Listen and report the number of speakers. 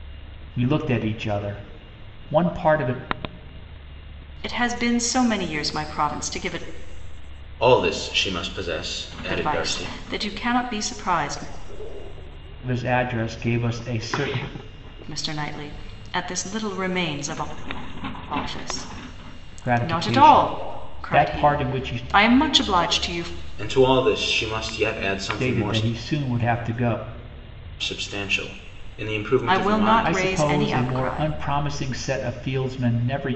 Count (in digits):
3